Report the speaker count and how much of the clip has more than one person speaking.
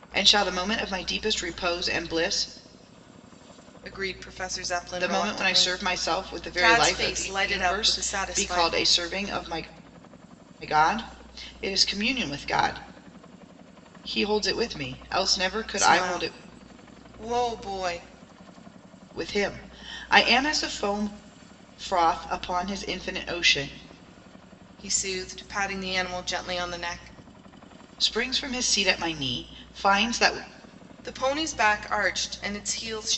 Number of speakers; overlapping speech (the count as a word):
two, about 11%